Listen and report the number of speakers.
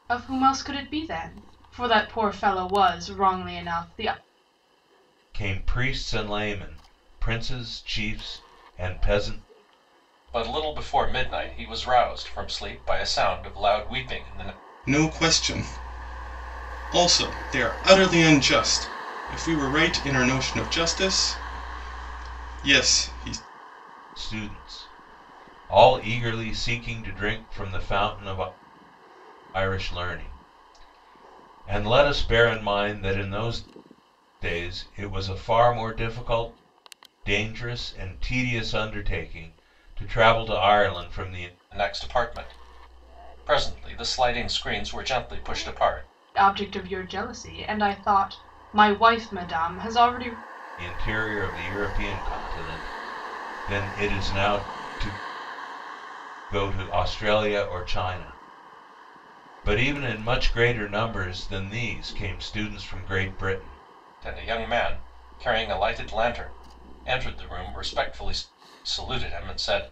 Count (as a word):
four